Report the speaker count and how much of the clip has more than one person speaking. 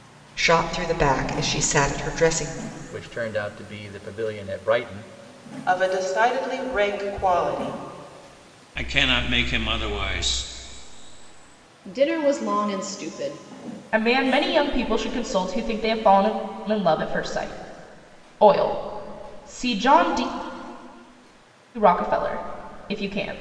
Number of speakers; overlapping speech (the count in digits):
6, no overlap